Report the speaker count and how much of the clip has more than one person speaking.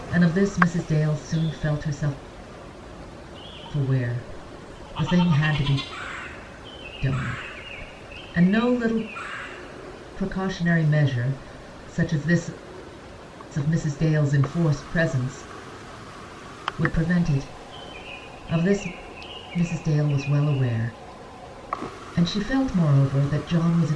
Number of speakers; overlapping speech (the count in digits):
1, no overlap